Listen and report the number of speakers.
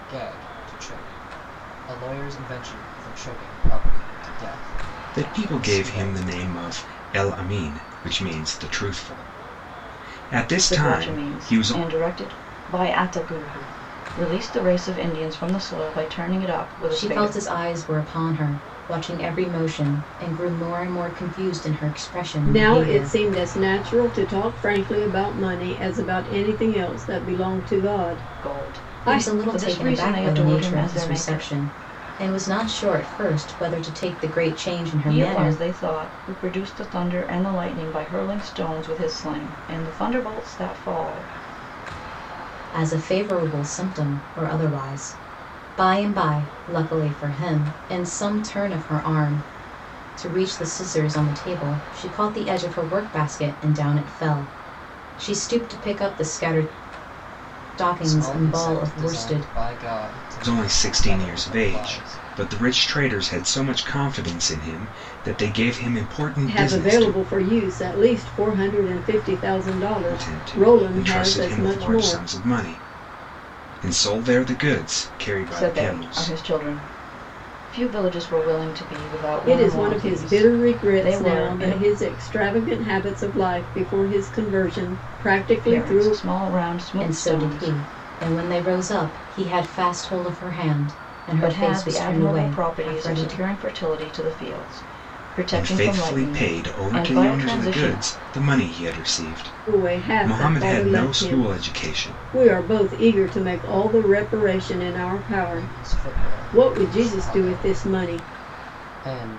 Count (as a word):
five